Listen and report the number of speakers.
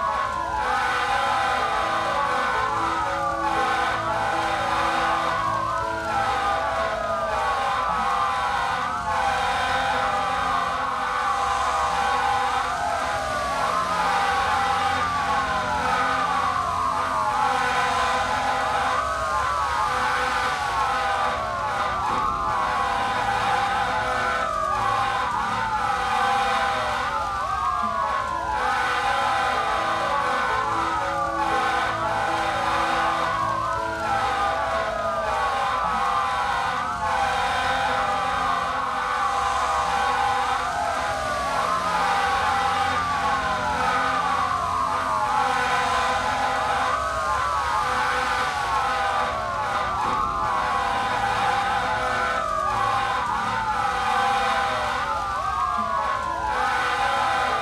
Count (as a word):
zero